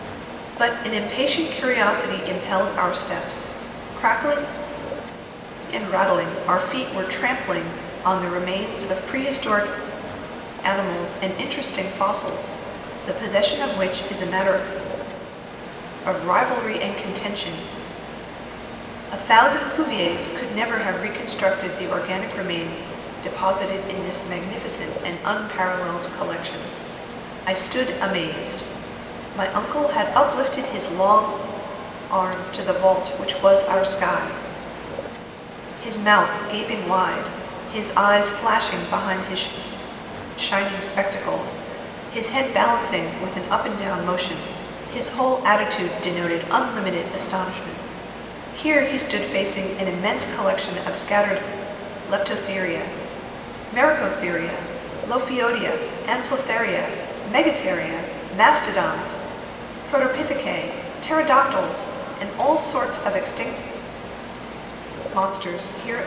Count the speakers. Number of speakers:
1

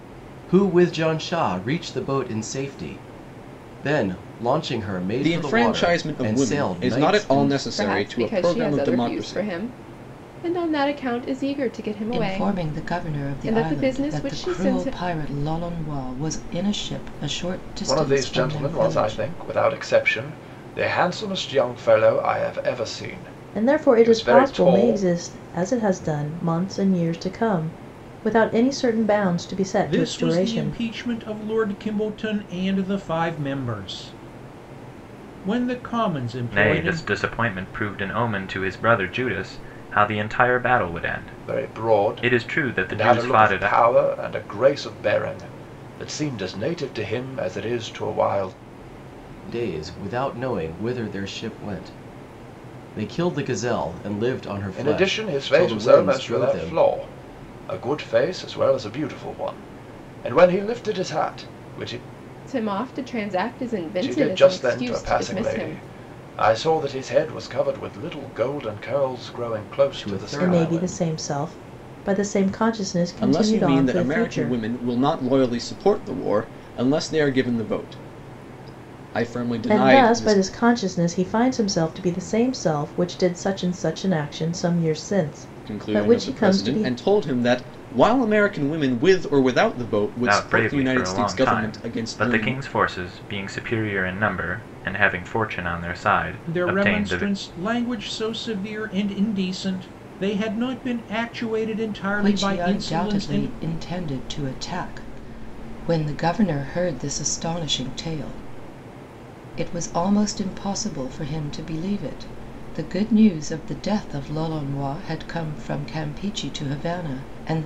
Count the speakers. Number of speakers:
8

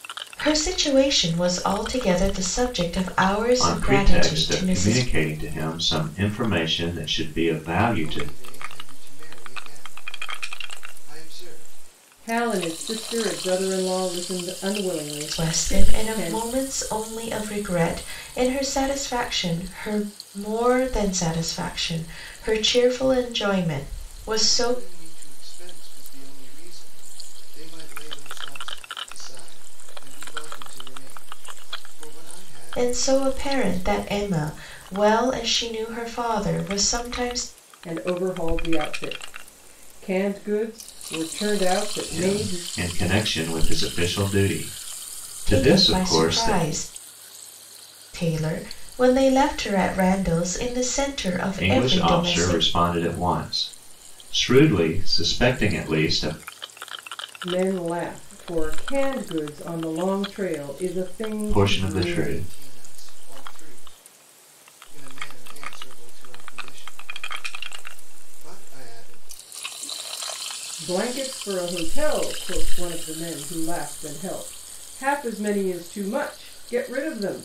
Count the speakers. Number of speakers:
4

